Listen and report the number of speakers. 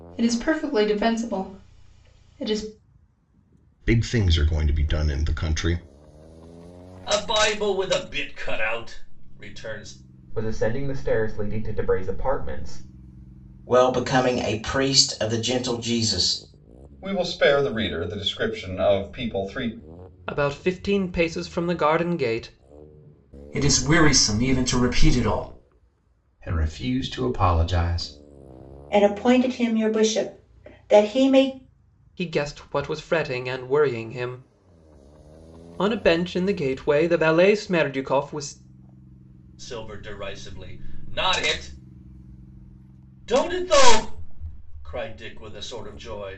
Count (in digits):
10